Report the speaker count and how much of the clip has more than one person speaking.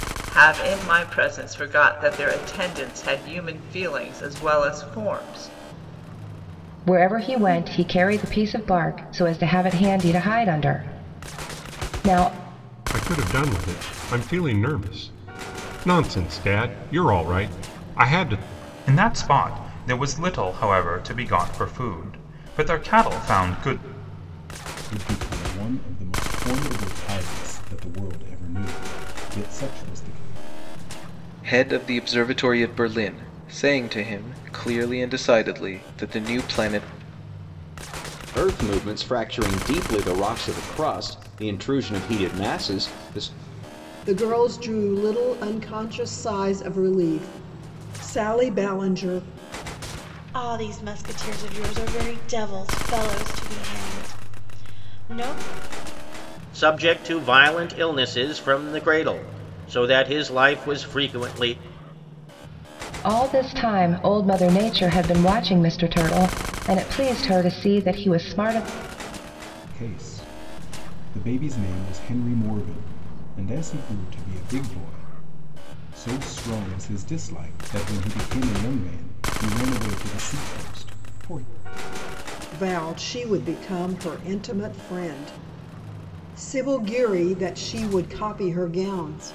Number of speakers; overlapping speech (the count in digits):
10, no overlap